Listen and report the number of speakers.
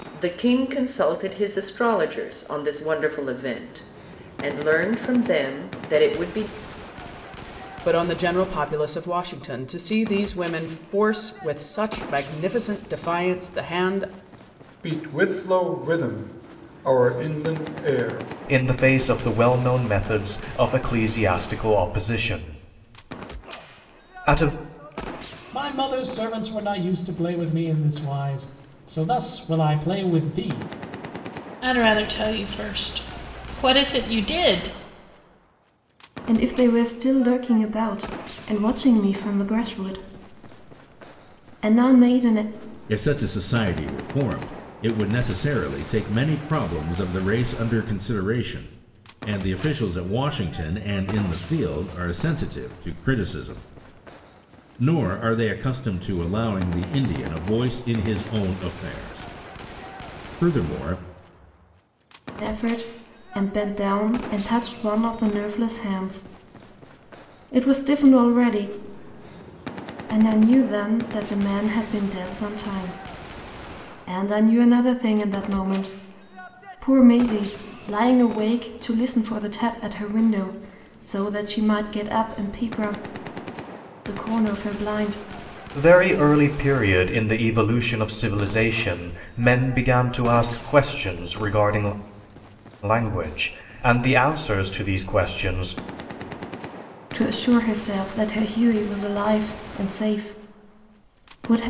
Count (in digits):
8